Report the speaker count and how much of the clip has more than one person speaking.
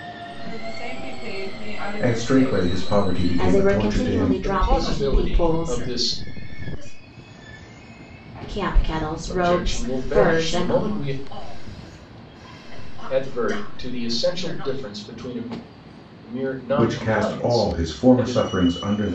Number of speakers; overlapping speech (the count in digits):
5, about 52%